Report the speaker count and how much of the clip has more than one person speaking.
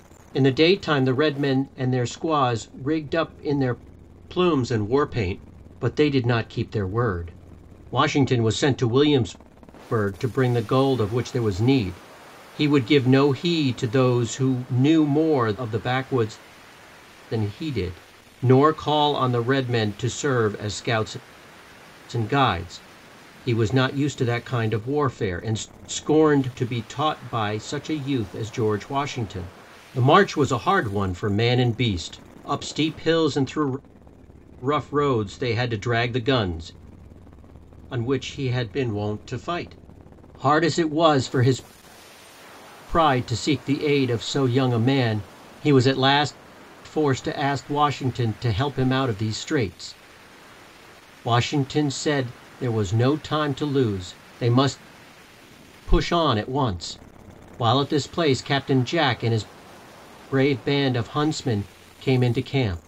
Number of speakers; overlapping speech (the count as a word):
one, no overlap